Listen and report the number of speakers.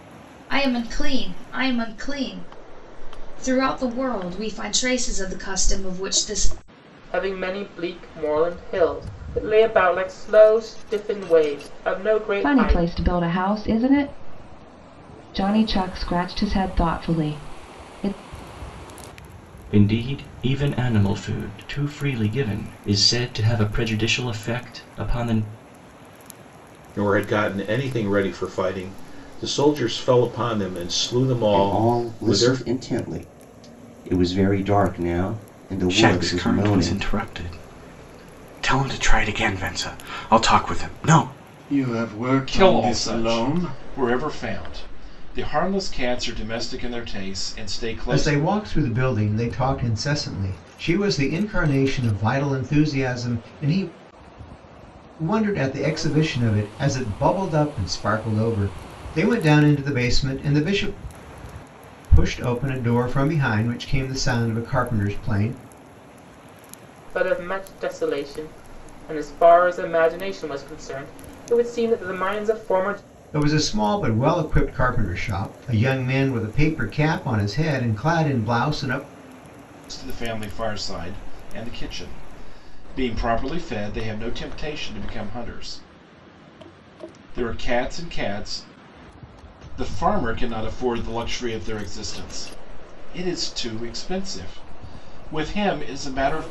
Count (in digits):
10